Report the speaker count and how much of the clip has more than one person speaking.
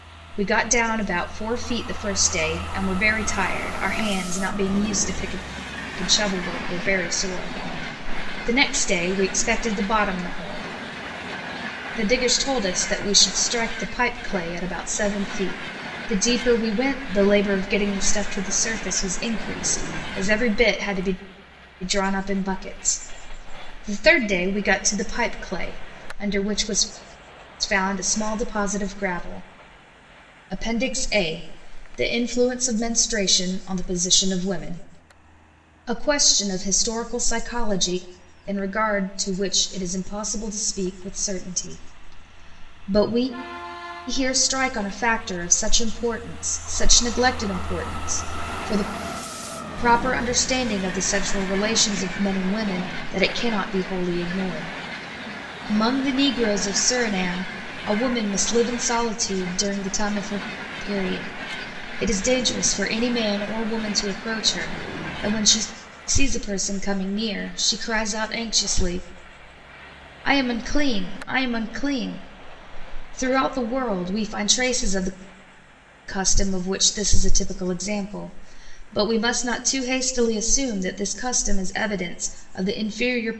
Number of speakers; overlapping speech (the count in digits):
1, no overlap